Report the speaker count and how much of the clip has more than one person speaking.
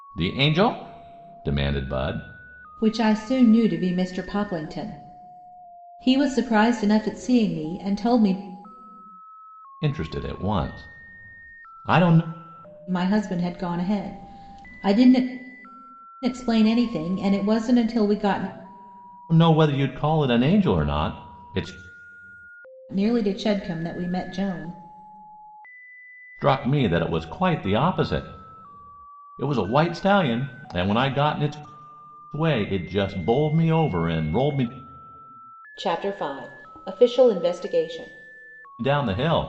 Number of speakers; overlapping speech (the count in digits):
2, no overlap